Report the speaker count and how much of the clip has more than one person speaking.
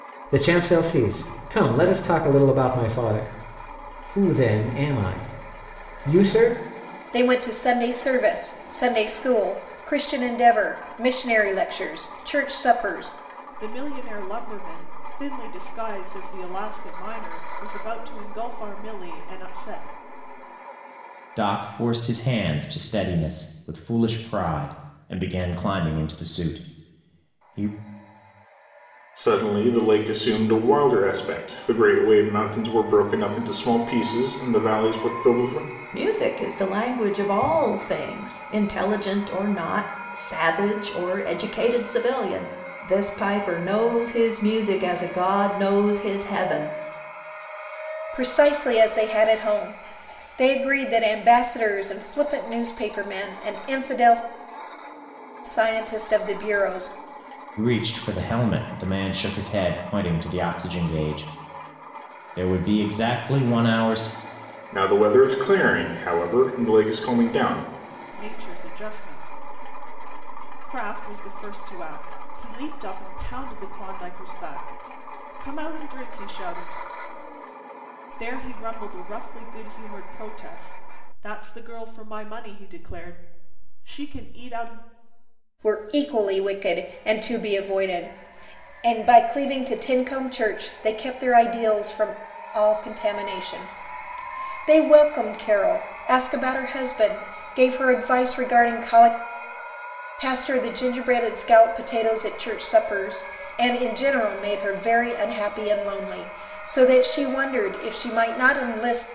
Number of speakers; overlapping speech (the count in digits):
6, no overlap